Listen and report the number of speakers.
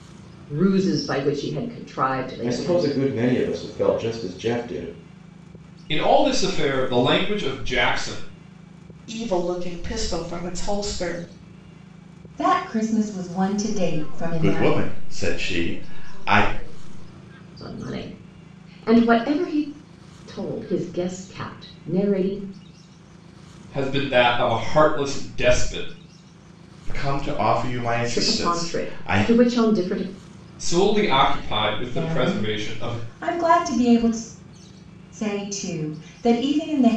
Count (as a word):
seven